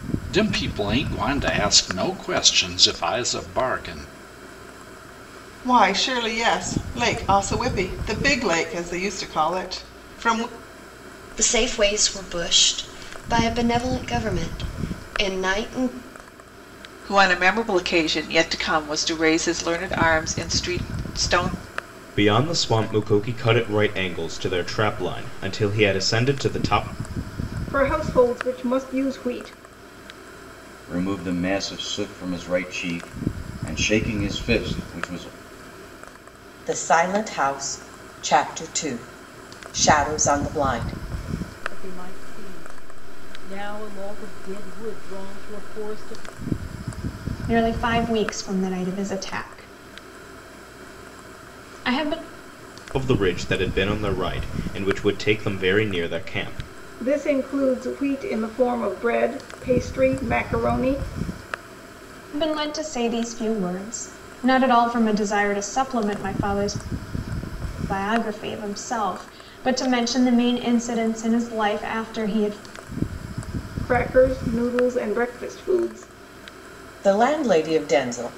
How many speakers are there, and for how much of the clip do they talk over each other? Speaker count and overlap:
10, no overlap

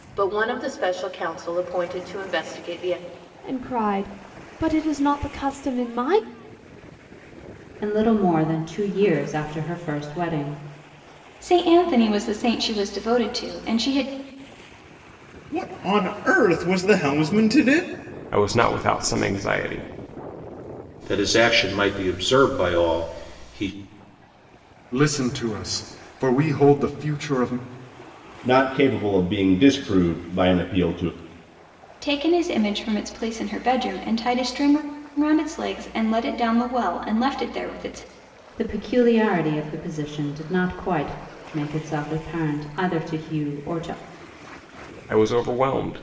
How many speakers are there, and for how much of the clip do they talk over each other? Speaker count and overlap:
9, no overlap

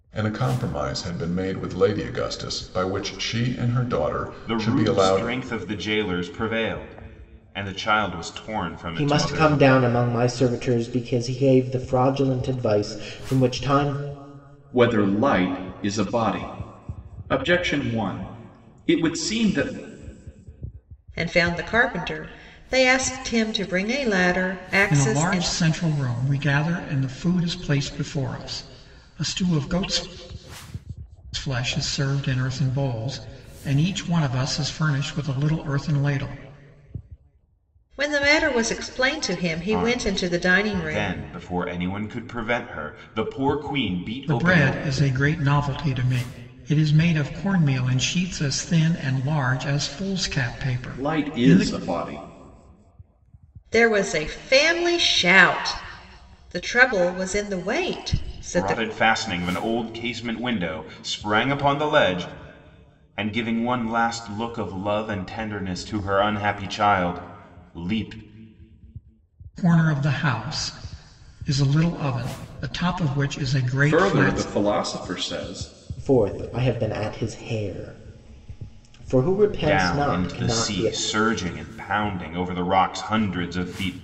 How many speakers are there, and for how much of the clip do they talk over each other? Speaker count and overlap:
6, about 9%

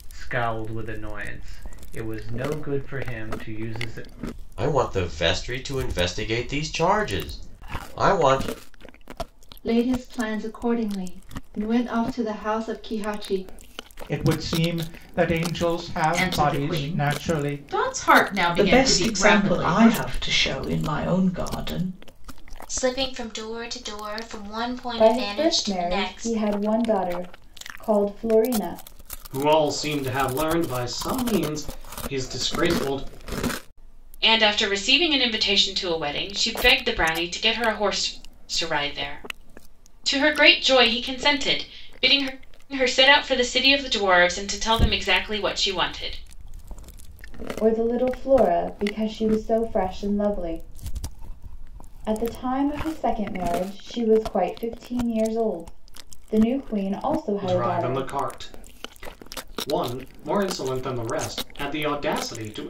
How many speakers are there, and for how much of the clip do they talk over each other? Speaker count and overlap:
10, about 8%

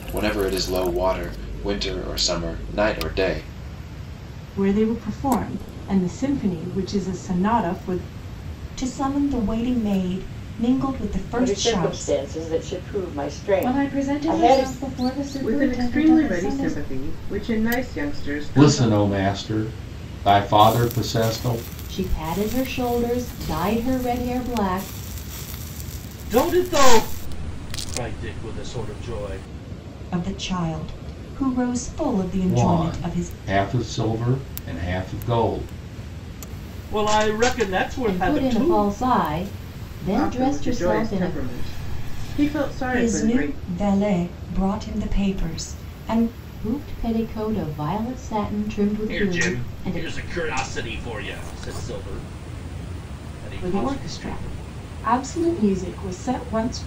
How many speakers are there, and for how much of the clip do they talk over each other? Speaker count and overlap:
9, about 17%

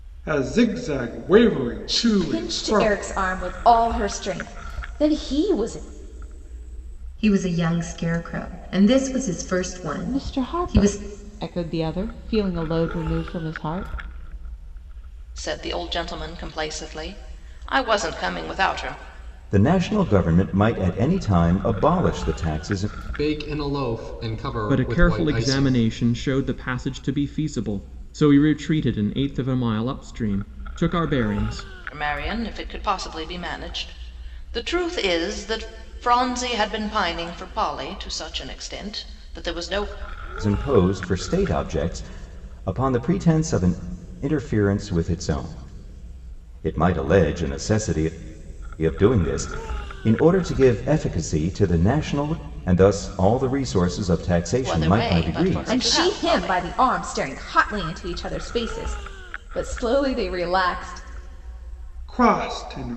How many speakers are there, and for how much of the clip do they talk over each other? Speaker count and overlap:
8, about 8%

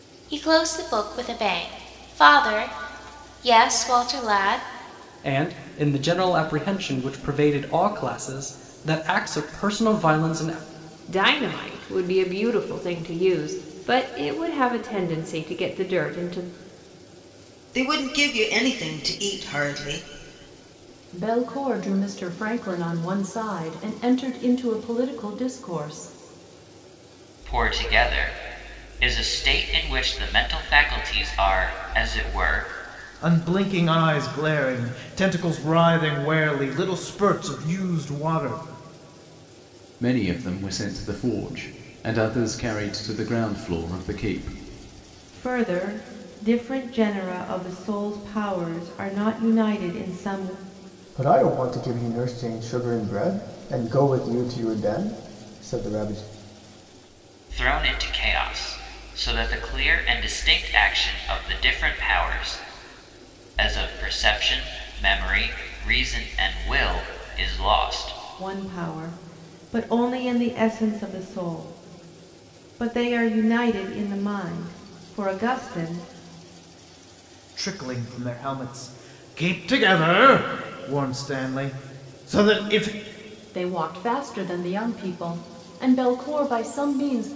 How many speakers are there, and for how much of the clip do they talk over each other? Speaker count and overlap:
10, no overlap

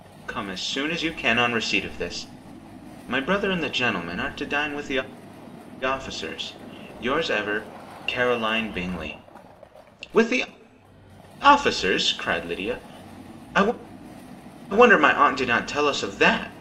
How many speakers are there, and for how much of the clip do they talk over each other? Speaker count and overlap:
1, no overlap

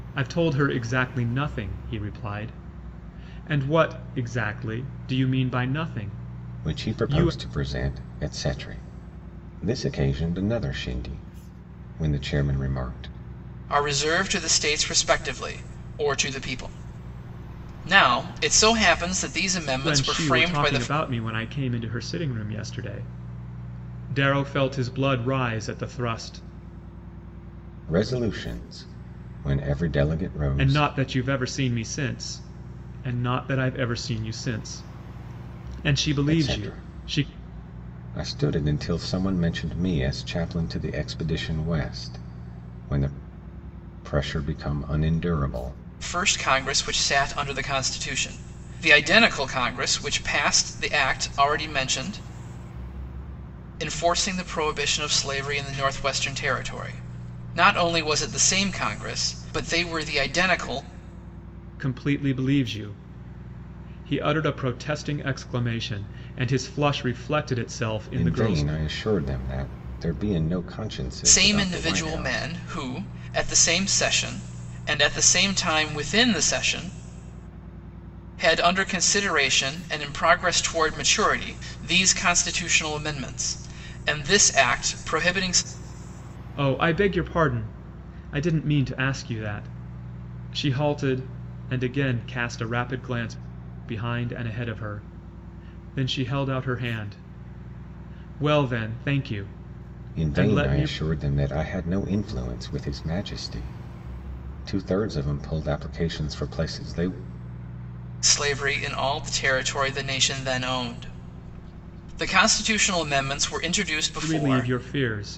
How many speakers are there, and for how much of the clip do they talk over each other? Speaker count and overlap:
3, about 6%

